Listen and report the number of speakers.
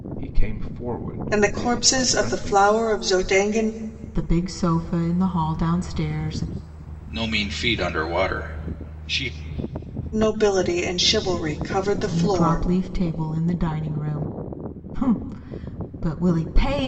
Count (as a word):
four